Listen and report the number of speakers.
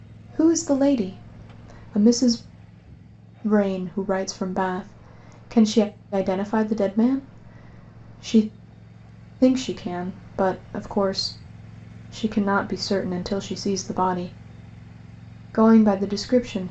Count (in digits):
1